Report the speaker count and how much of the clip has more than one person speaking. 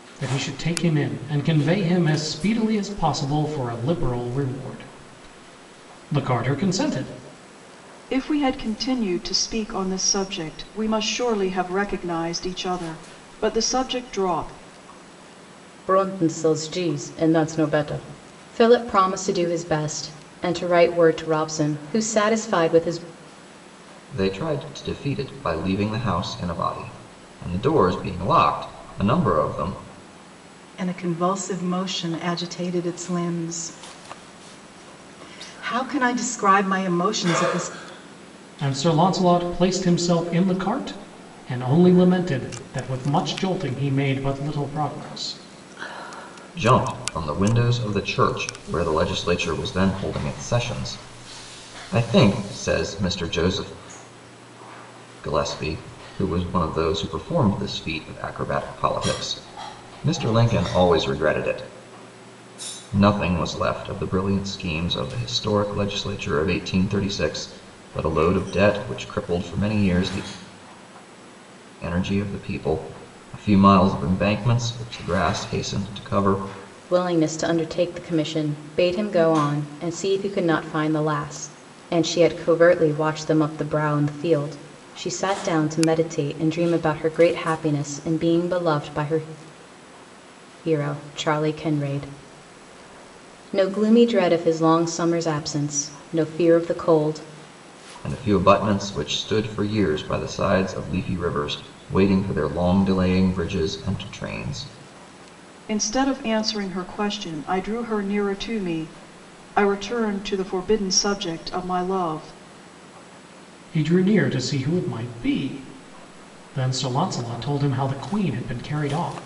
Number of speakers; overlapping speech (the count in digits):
5, no overlap